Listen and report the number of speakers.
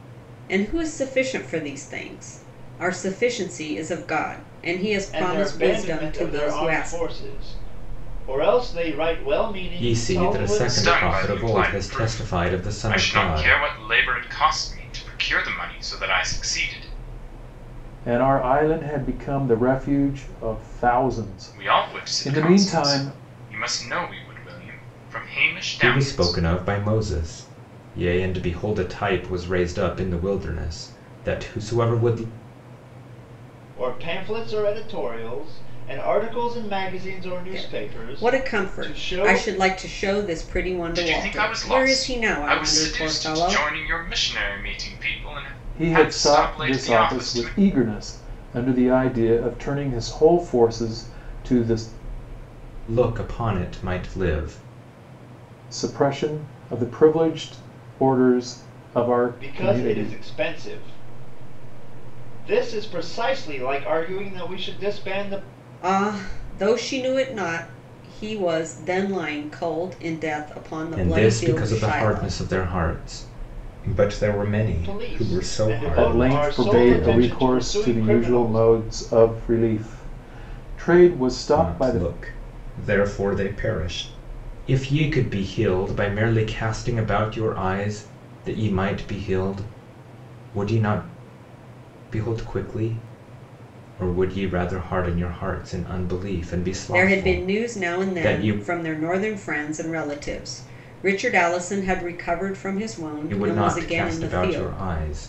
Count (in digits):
5